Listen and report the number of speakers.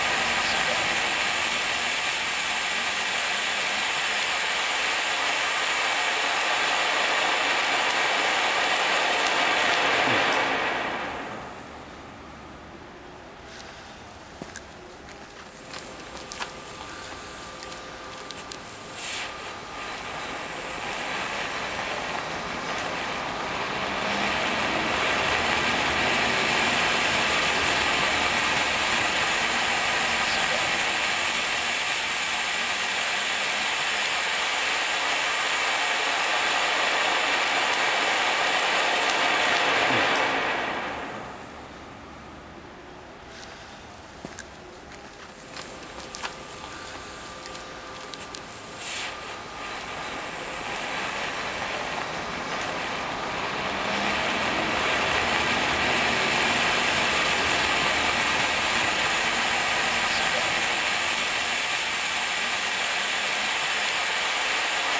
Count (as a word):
zero